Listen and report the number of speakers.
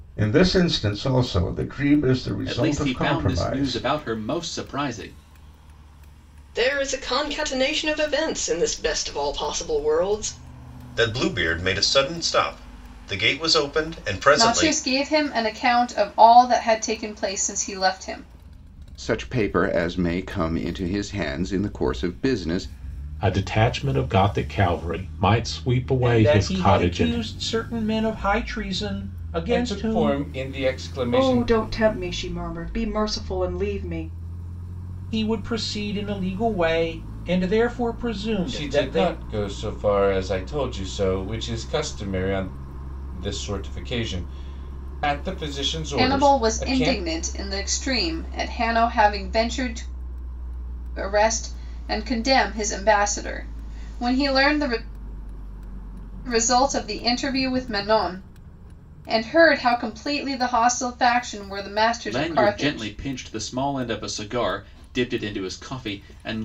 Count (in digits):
10